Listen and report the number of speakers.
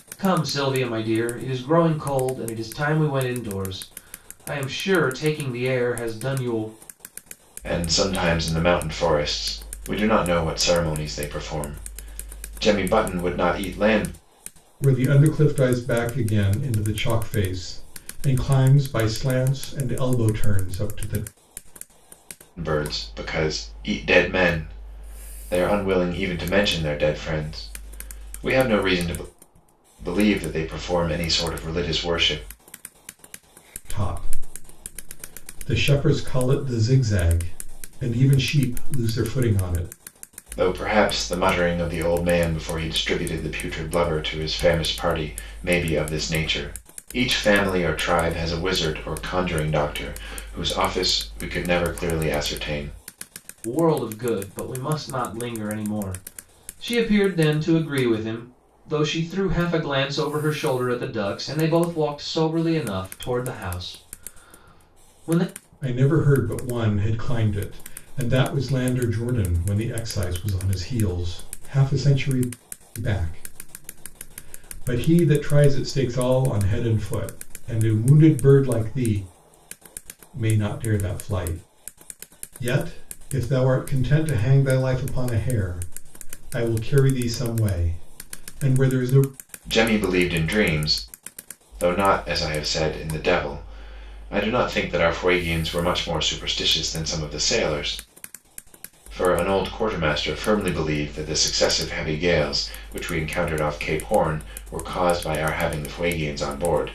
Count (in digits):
3